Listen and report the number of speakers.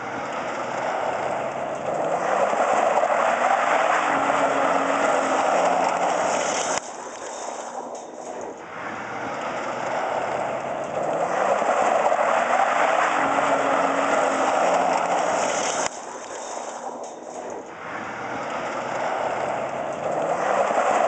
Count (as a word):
zero